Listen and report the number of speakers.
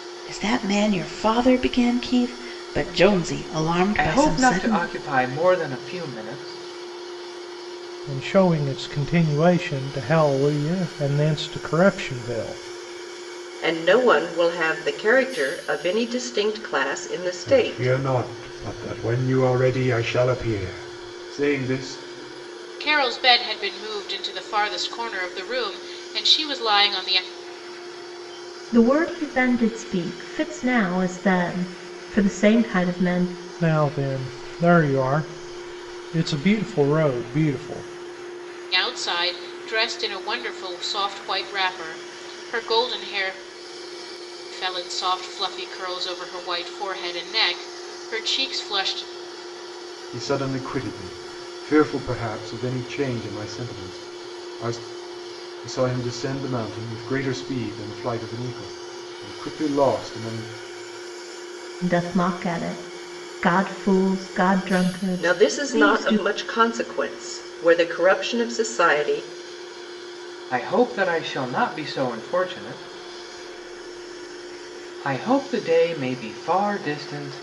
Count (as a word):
seven